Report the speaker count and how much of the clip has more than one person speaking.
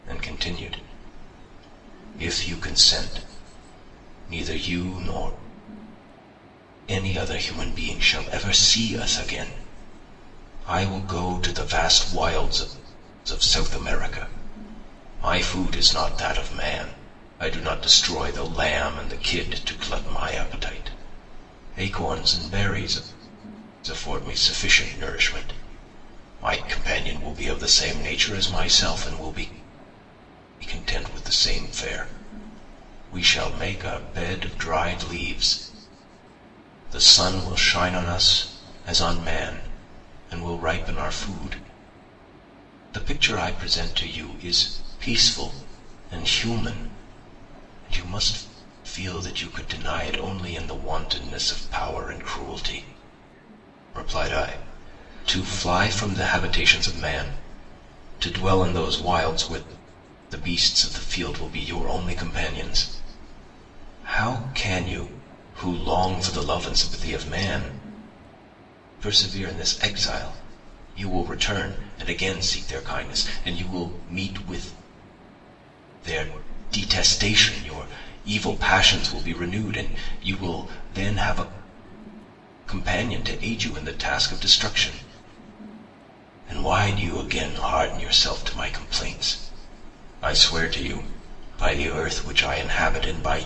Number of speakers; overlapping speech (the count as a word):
one, no overlap